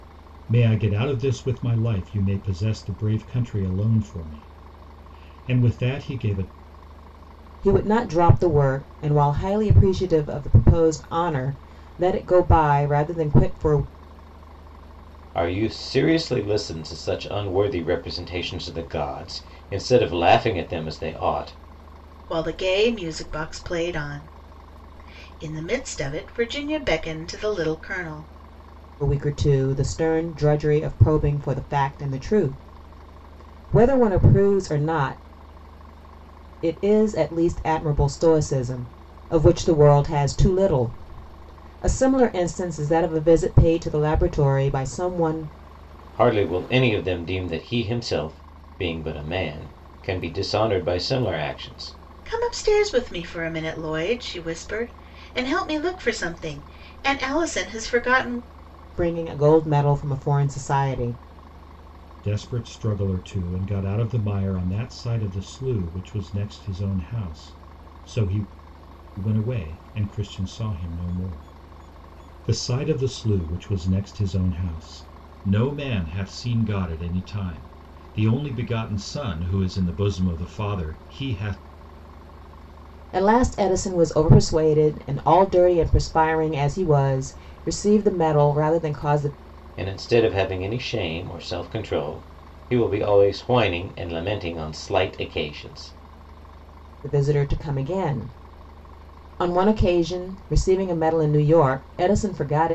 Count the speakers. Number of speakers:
4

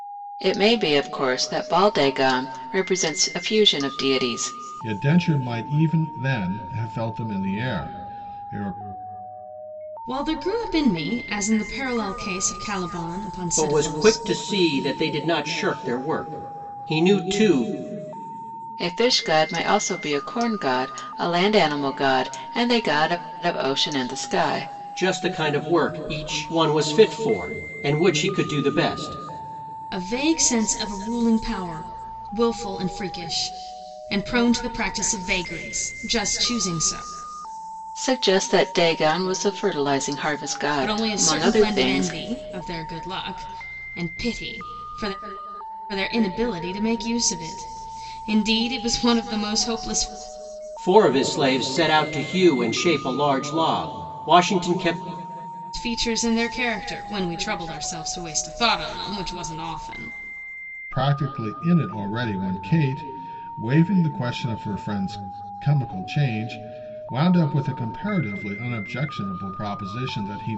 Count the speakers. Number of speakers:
4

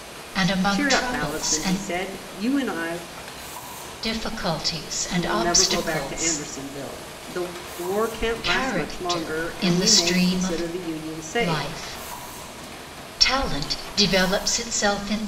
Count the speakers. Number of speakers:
2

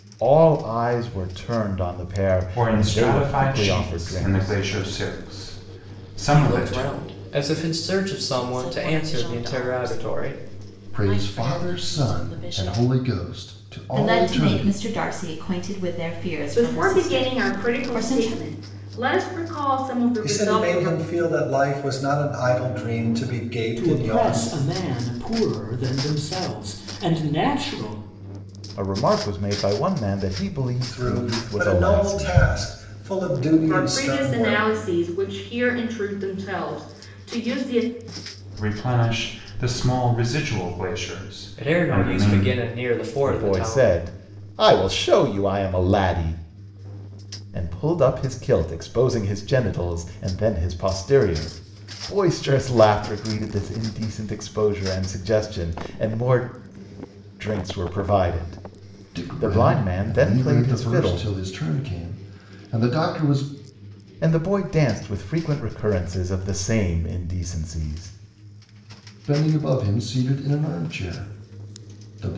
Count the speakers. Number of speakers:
9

